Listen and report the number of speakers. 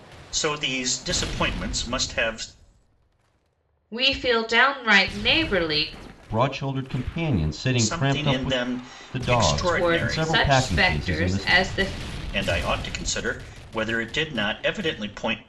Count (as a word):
three